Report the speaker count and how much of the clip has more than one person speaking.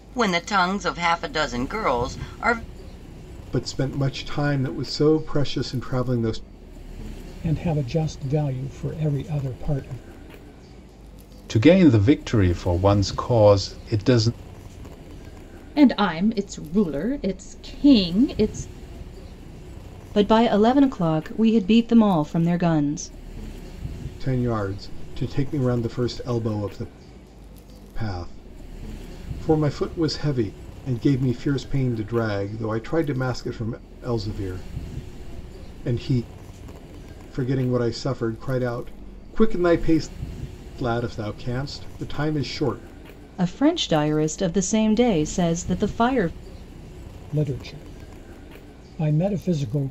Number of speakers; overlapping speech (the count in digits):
6, no overlap